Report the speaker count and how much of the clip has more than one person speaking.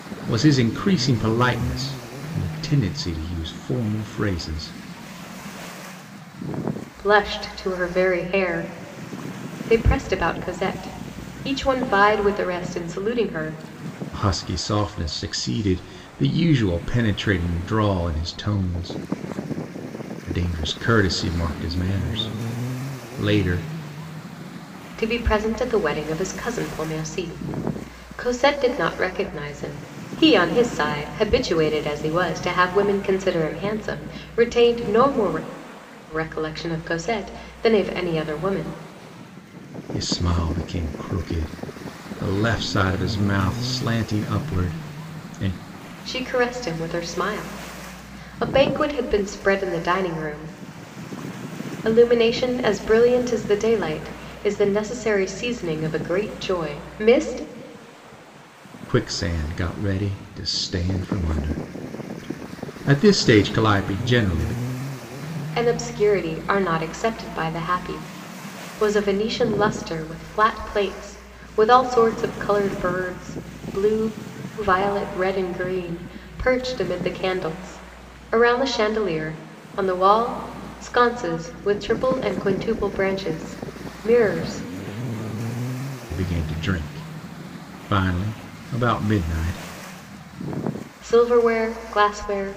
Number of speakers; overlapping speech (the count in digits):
2, no overlap